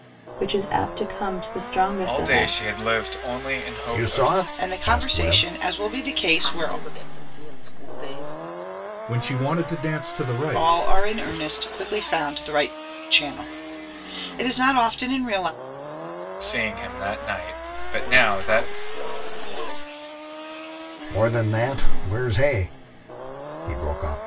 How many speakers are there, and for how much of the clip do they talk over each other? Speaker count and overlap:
six, about 18%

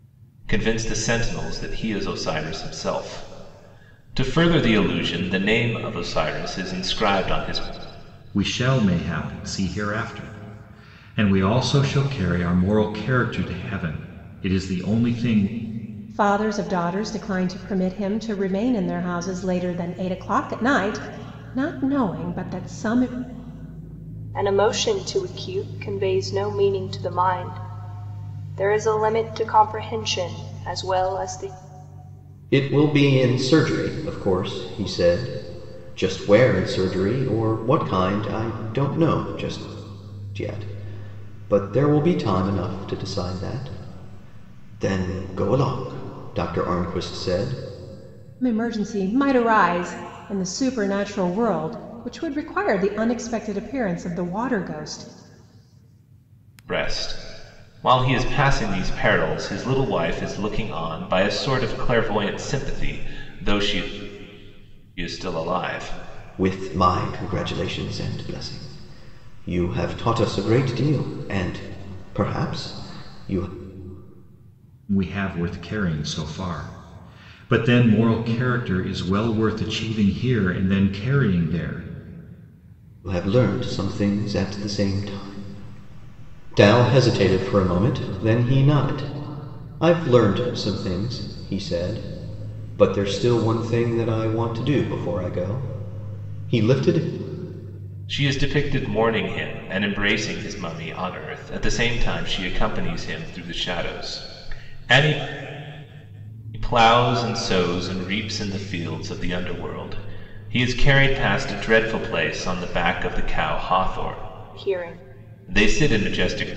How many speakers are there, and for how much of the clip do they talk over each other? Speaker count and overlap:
five, no overlap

